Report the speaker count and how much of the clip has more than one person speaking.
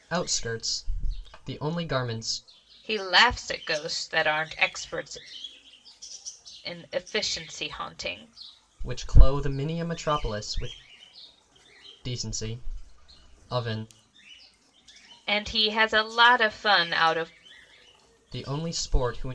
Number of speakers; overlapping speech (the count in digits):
2, no overlap